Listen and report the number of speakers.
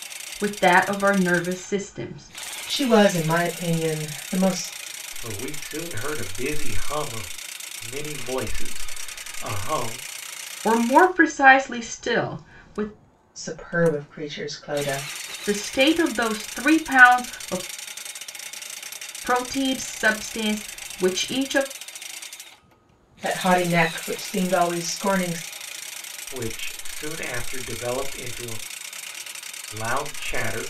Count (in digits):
3